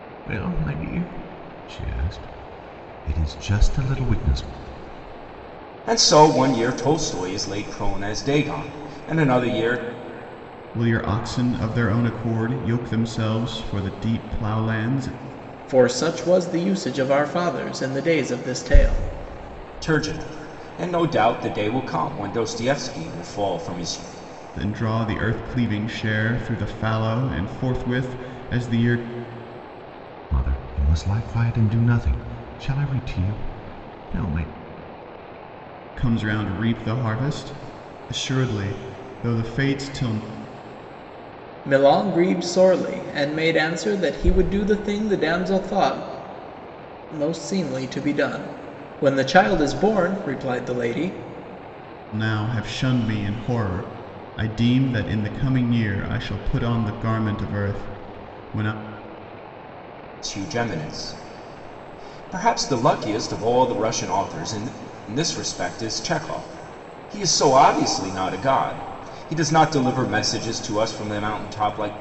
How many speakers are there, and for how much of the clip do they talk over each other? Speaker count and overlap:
4, no overlap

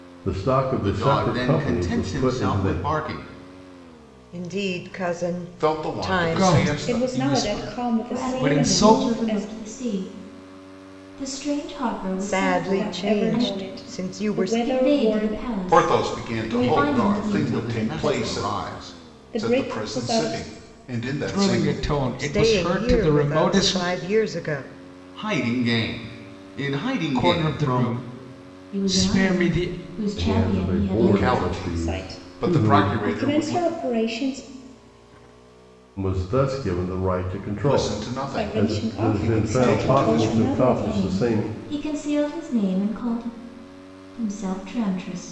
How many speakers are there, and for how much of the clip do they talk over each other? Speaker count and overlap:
7, about 55%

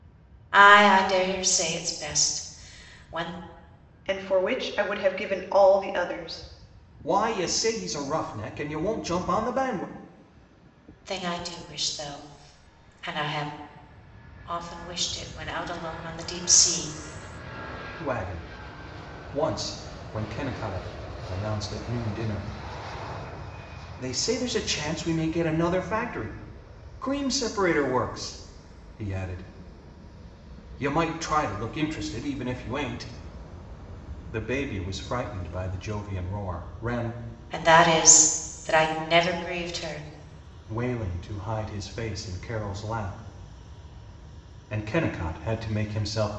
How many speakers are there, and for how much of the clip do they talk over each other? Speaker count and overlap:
3, no overlap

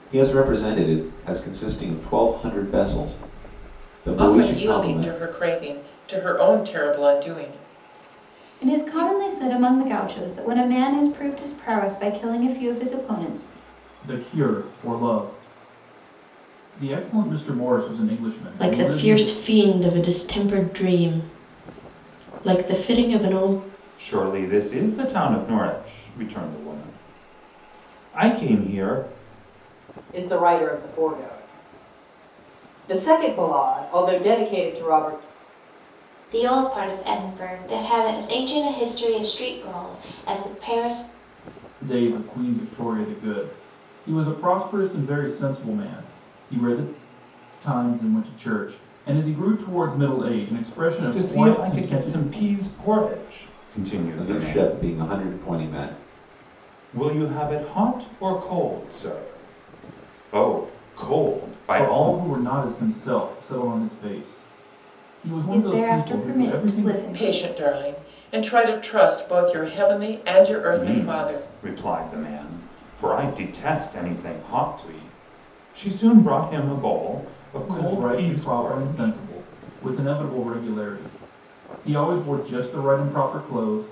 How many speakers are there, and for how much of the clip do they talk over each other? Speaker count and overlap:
8, about 11%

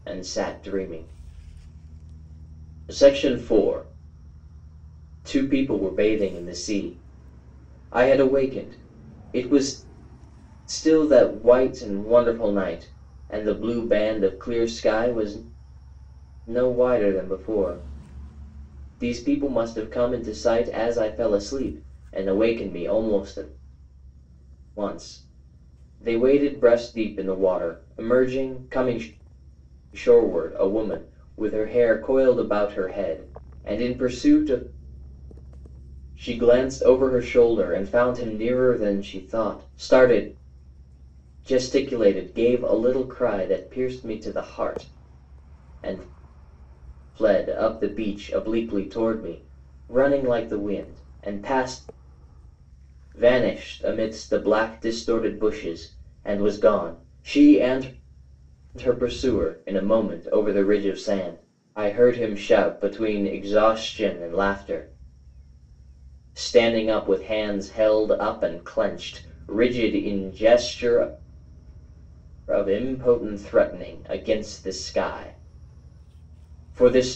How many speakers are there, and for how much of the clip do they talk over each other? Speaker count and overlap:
1, no overlap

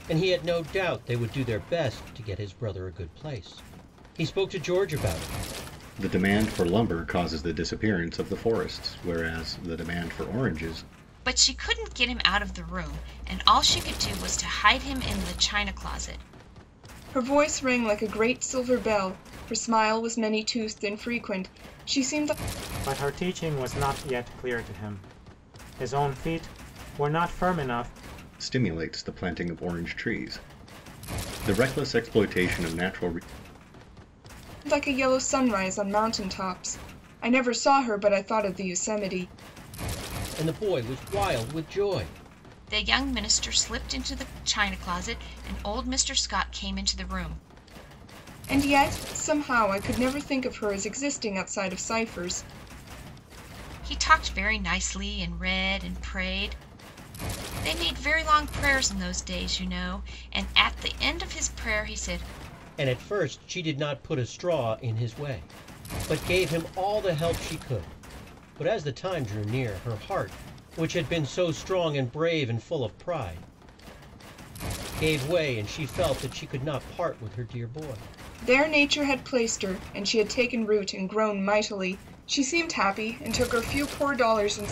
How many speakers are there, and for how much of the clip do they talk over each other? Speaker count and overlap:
5, no overlap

